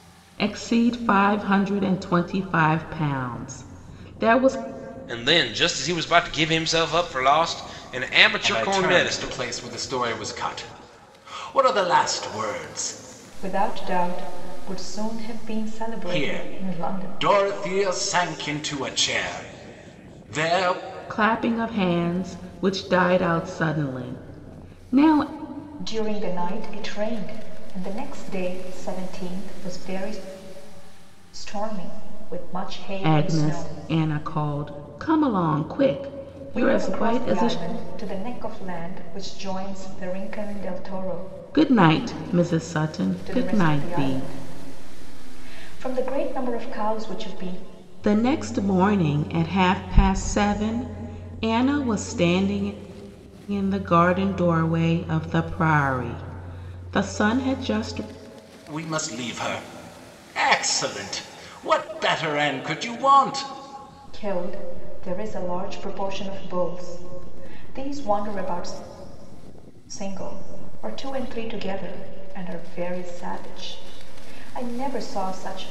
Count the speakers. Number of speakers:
4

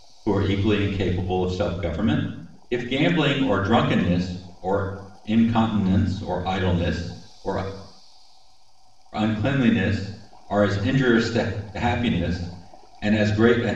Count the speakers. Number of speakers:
1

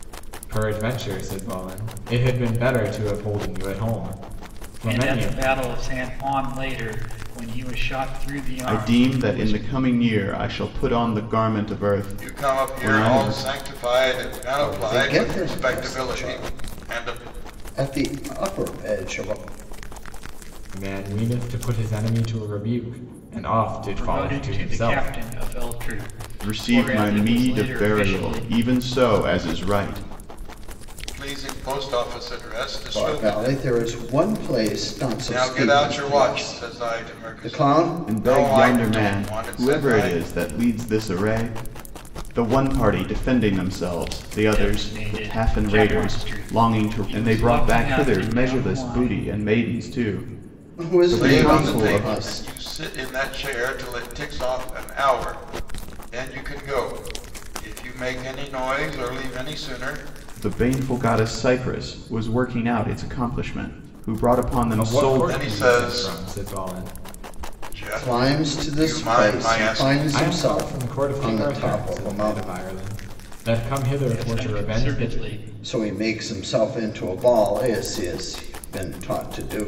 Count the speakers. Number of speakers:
5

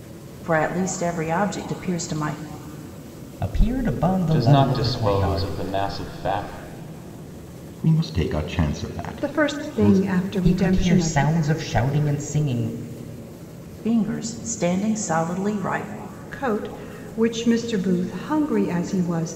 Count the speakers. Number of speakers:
5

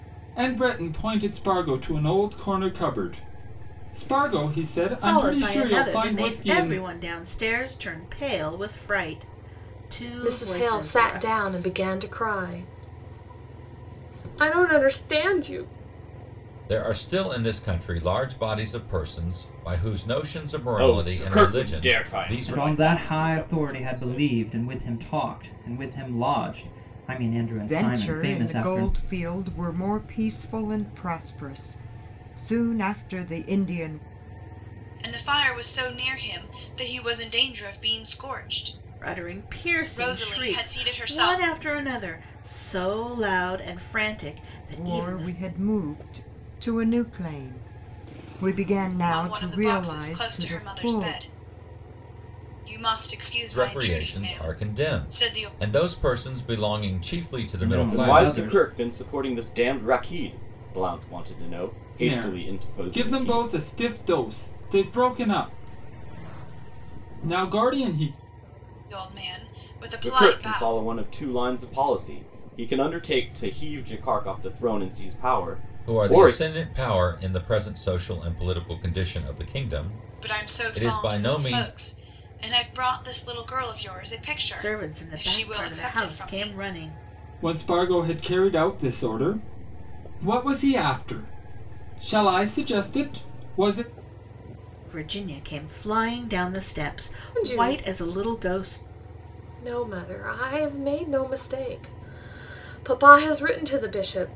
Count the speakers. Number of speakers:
8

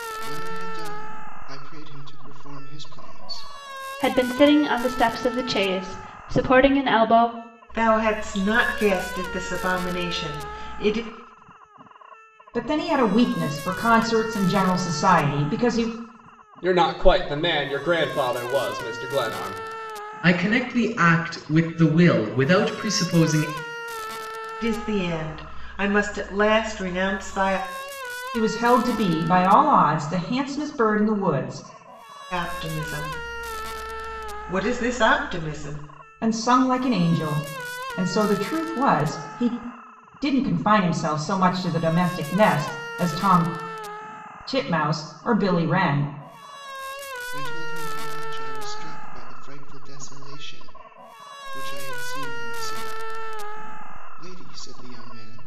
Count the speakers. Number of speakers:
6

